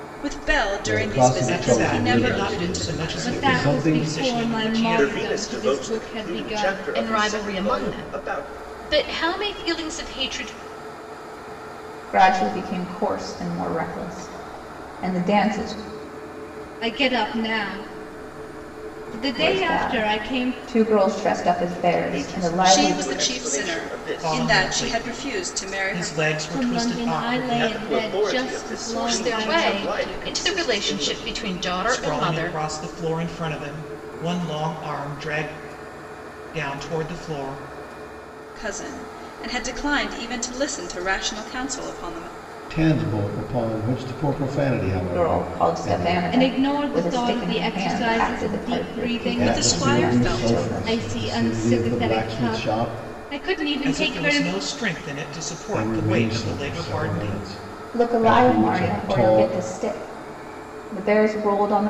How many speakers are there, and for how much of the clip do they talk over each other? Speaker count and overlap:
7, about 50%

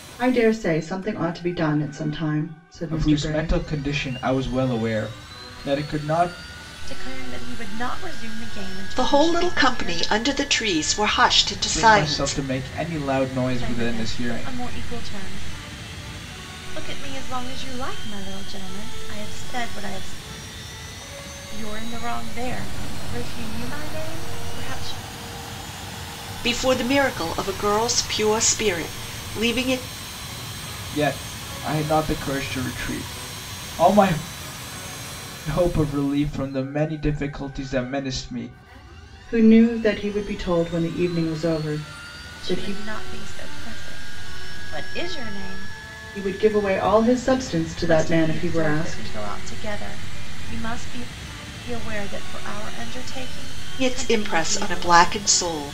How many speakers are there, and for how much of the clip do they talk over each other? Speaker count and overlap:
4, about 12%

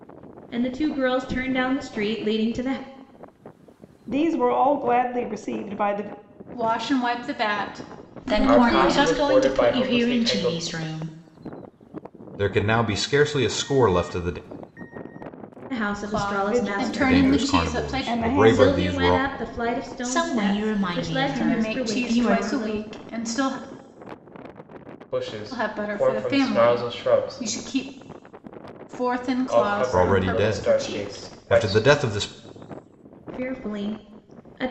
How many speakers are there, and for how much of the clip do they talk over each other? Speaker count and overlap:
7, about 36%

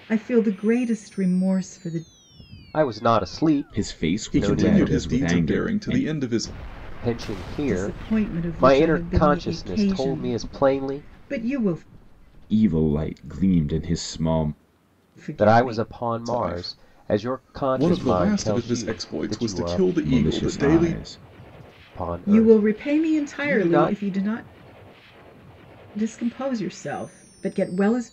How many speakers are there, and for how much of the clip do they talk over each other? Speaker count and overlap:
4, about 45%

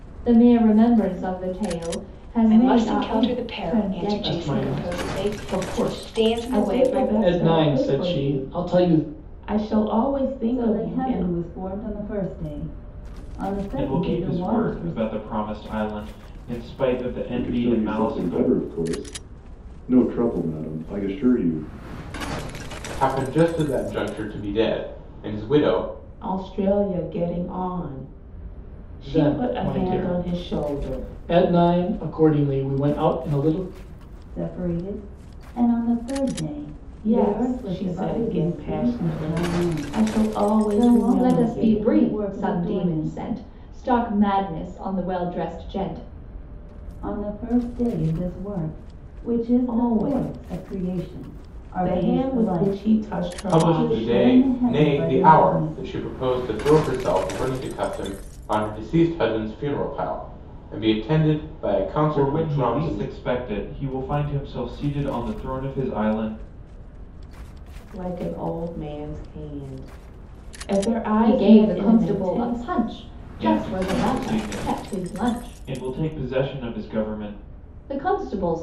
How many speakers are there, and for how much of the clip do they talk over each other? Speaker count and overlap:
8, about 37%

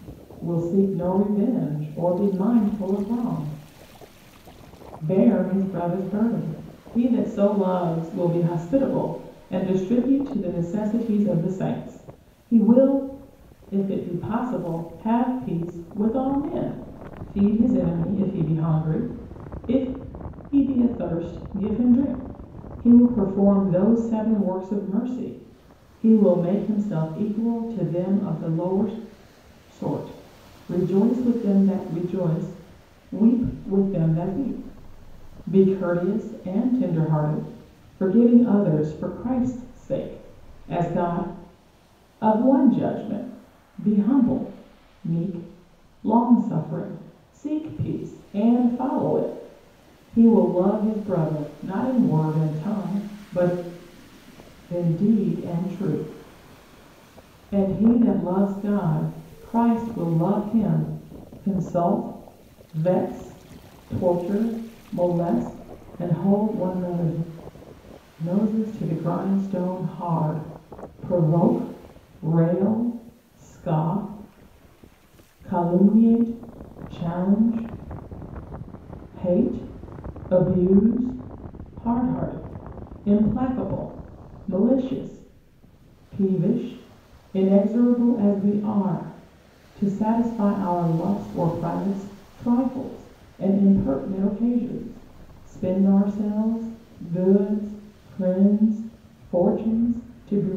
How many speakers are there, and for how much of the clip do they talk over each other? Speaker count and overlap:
1, no overlap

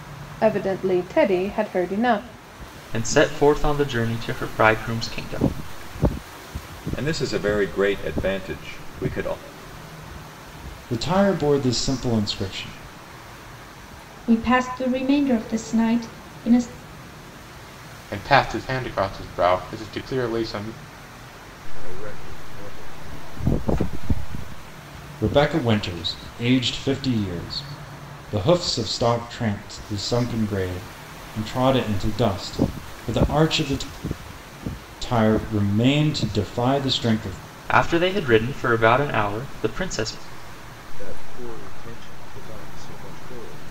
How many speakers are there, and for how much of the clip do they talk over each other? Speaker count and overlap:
7, no overlap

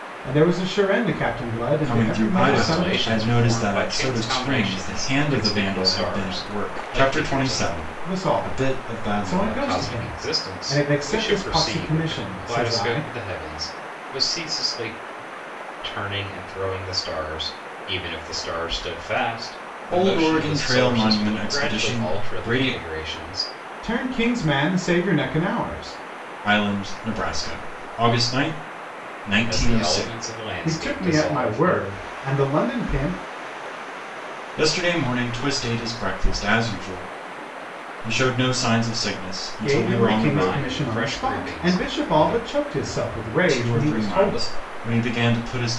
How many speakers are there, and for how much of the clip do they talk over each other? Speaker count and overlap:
3, about 43%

